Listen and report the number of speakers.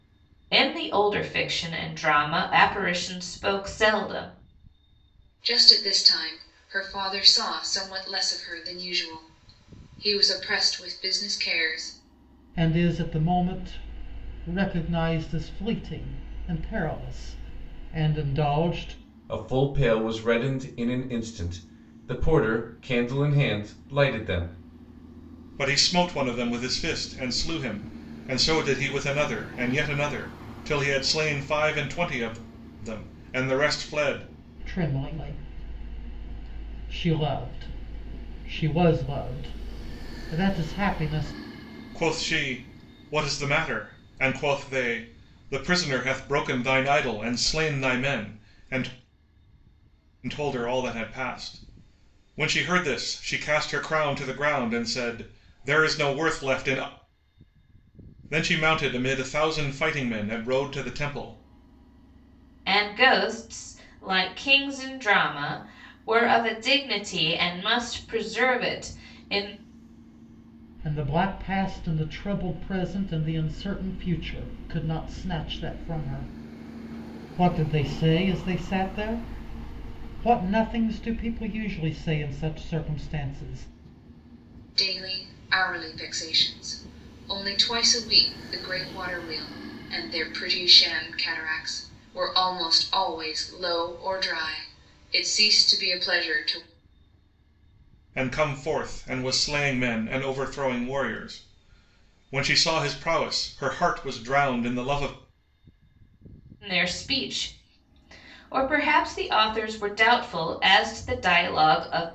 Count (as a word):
five